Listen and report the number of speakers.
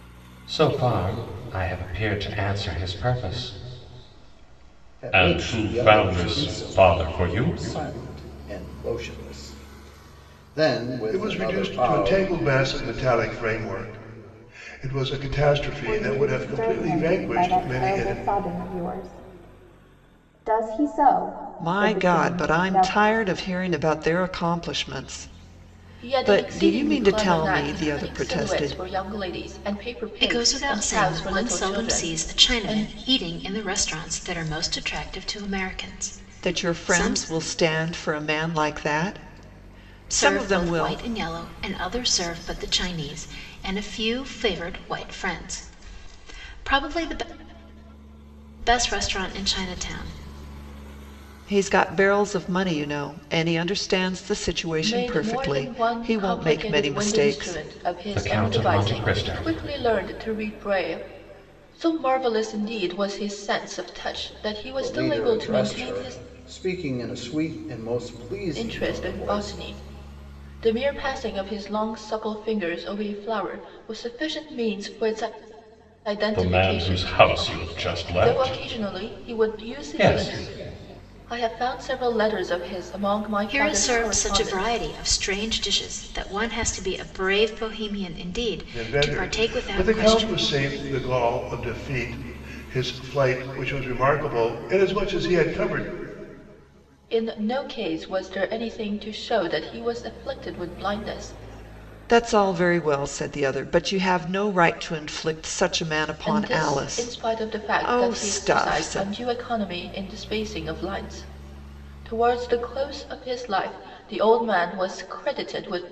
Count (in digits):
7